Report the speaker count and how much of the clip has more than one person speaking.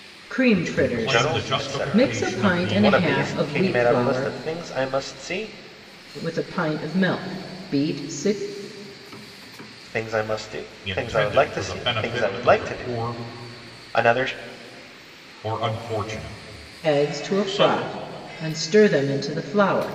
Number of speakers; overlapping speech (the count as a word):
three, about 35%